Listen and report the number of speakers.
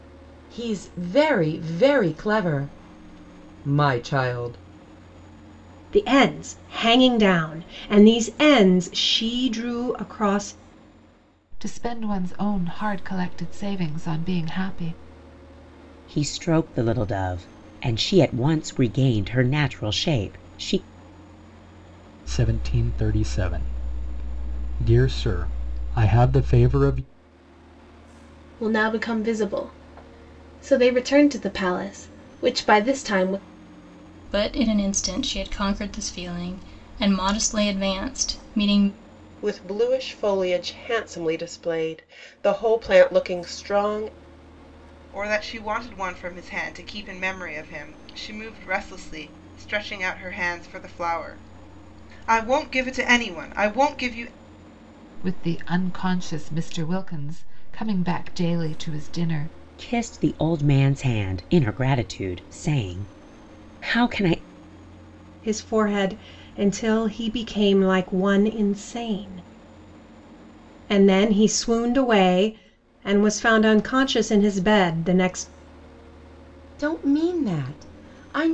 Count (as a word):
nine